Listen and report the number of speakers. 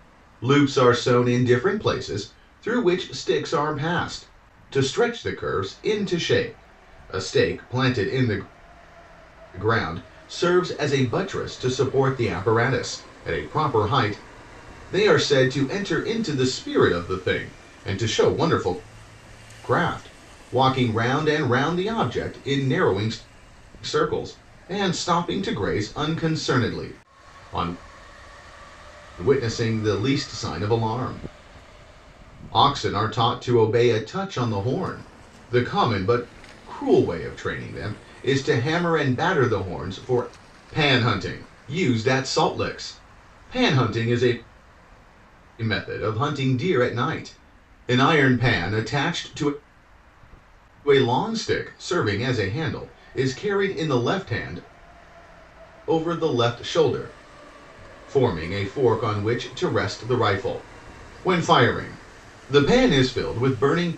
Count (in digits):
1